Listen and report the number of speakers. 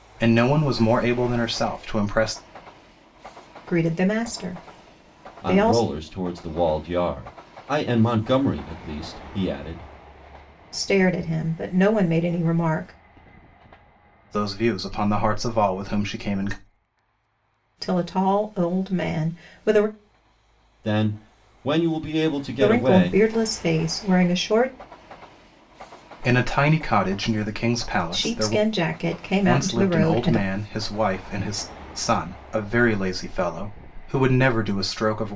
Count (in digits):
3